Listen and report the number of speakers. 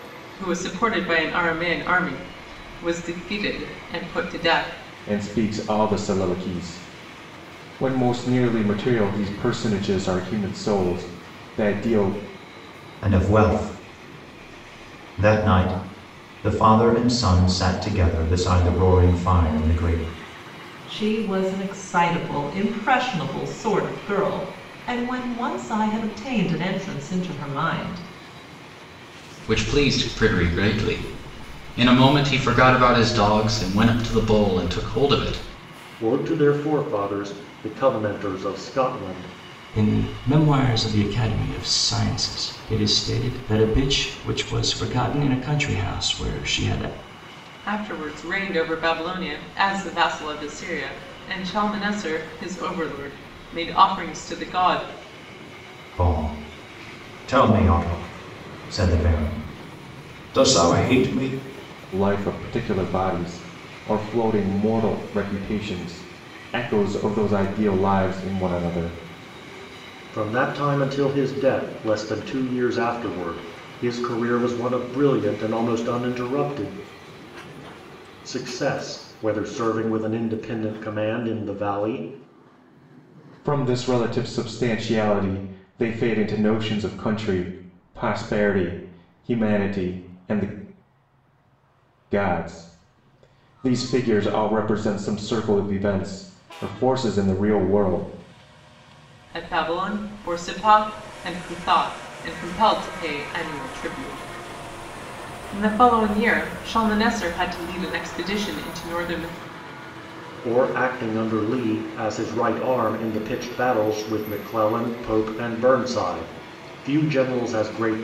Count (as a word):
seven